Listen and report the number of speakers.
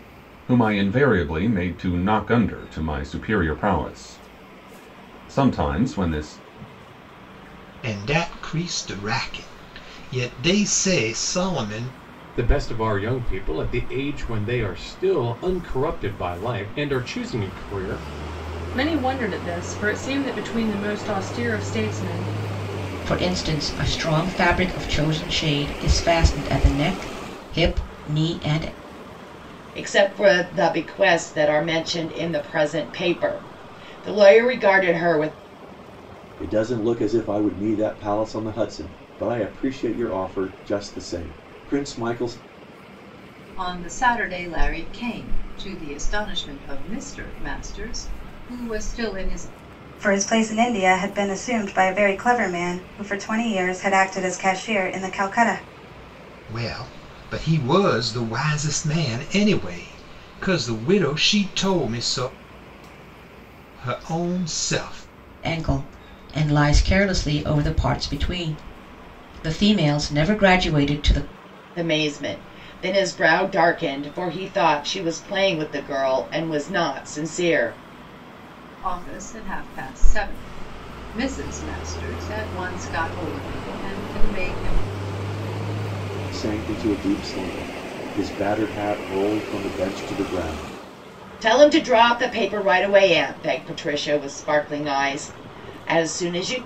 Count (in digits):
9